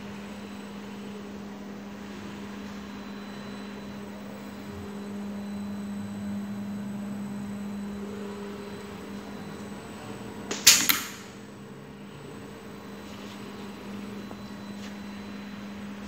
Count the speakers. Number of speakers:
0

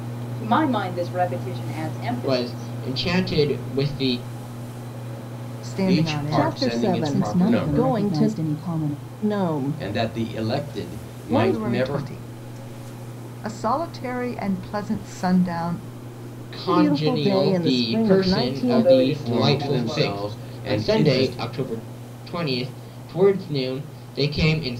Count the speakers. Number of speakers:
6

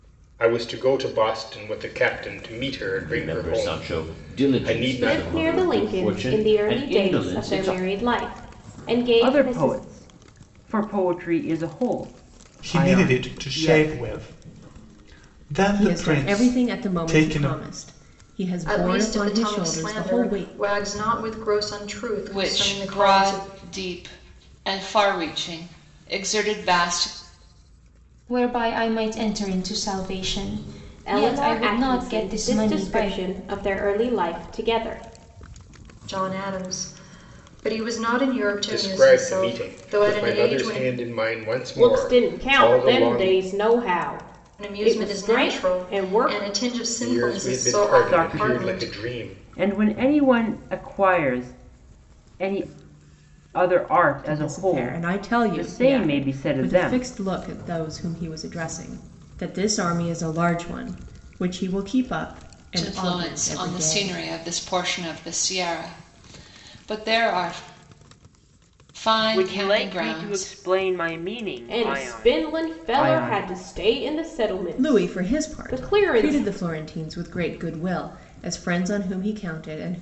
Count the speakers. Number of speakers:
9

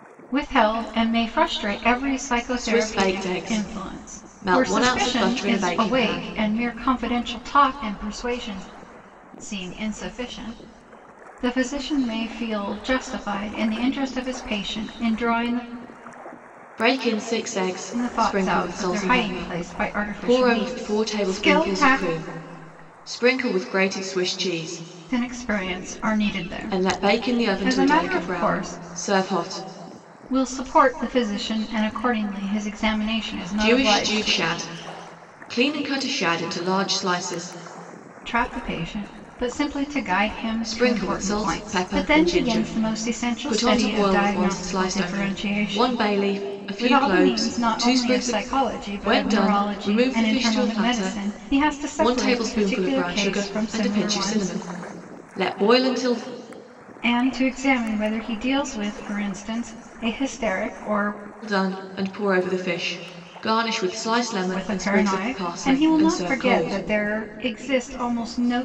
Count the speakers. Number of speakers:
2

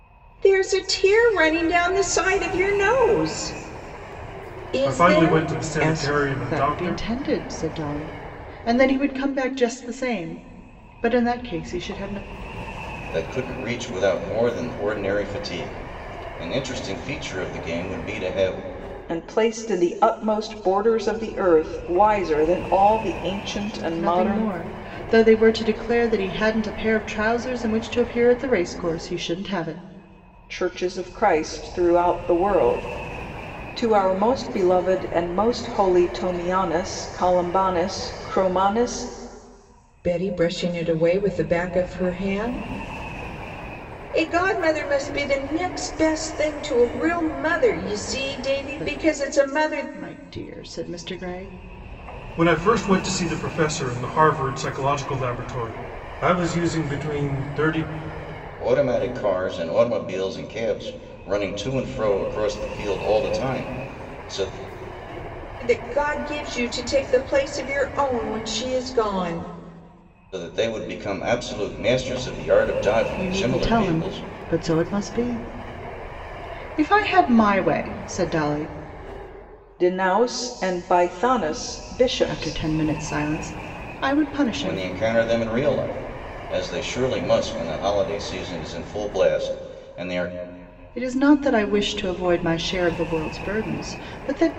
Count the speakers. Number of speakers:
5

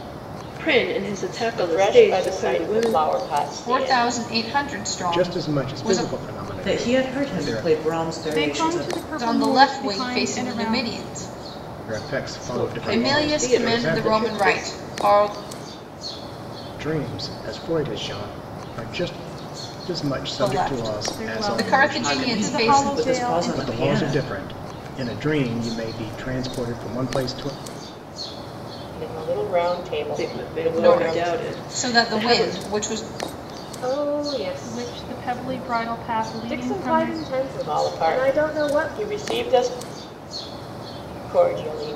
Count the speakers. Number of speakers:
7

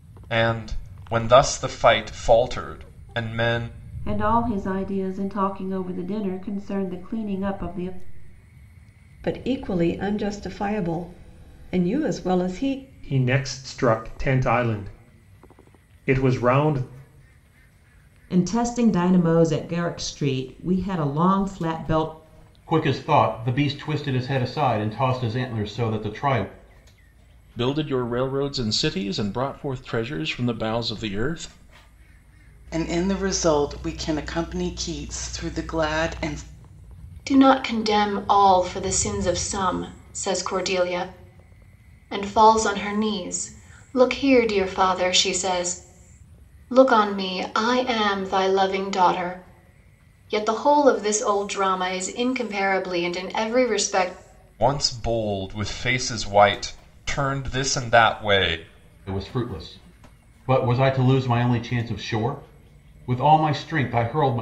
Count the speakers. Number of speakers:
9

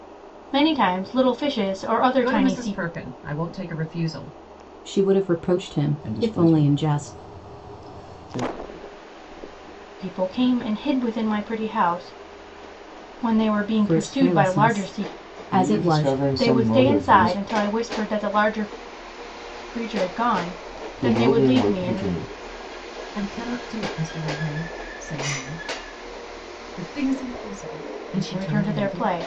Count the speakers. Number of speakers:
4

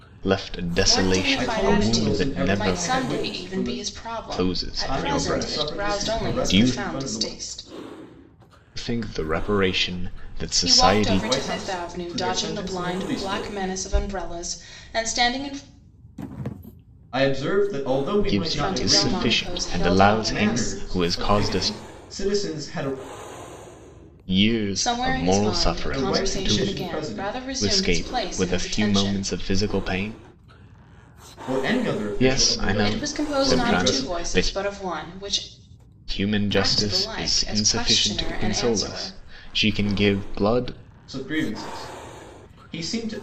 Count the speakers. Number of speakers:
3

